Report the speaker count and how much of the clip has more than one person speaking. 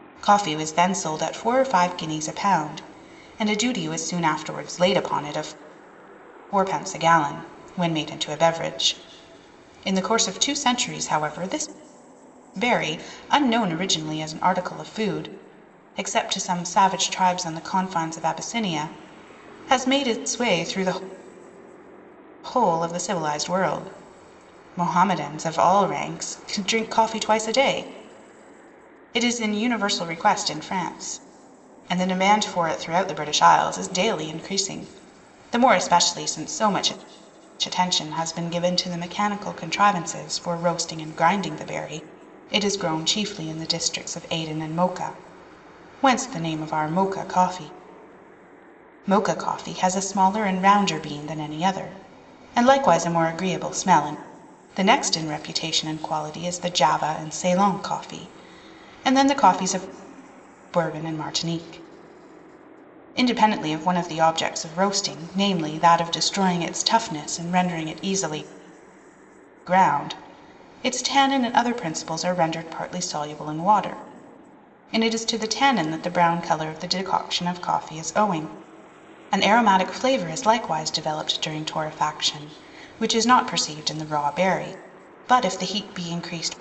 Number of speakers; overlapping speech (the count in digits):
1, no overlap